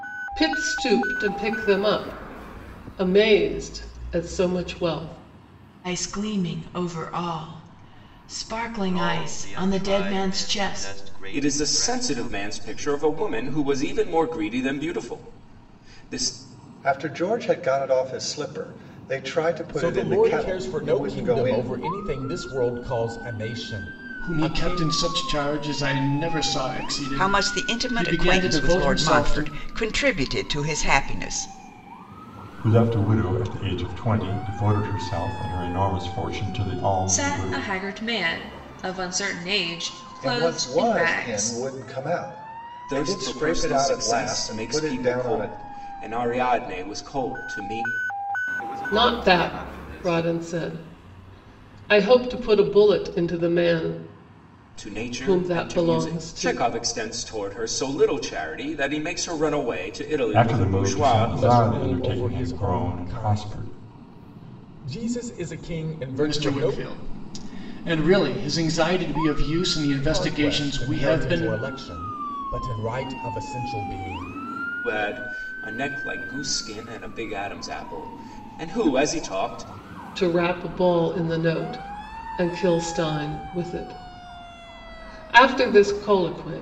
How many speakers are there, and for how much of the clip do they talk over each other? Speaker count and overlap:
ten, about 27%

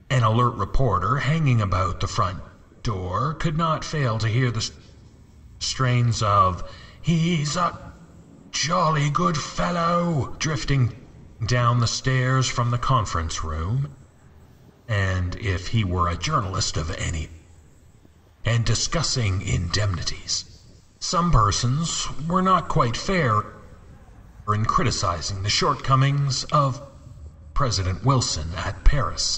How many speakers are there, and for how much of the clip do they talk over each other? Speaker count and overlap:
one, no overlap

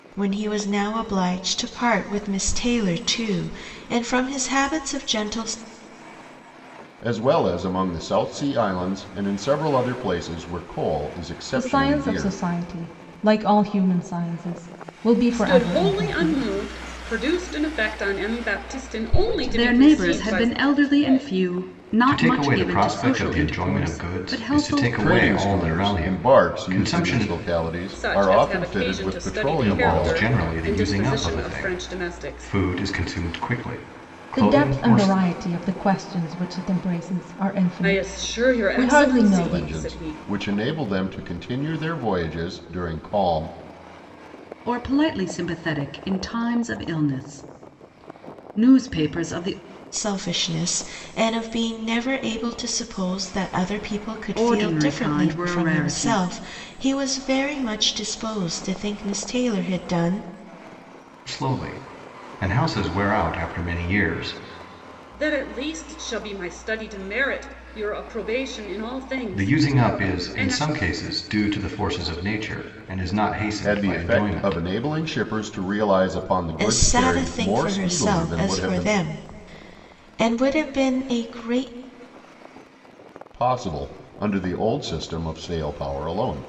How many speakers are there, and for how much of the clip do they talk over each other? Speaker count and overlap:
seven, about 28%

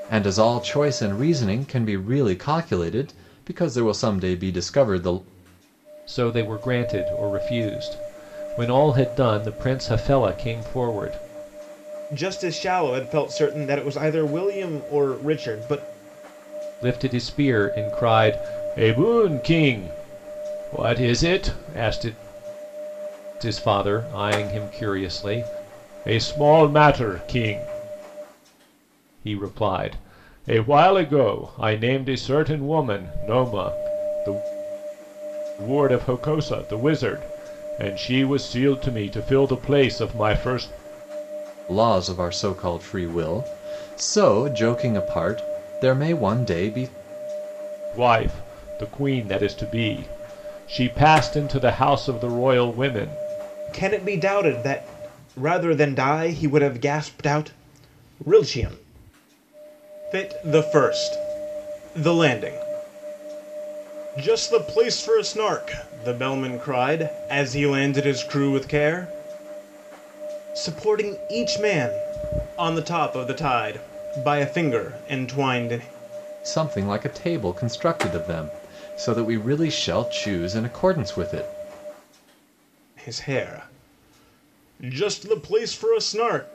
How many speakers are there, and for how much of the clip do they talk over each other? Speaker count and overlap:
three, no overlap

